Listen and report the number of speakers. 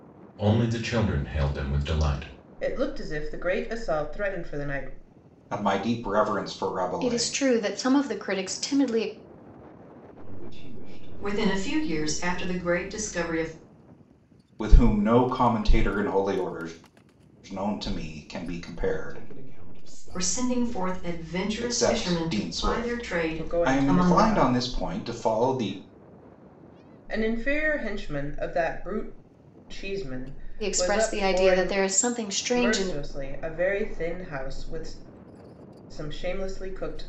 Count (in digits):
6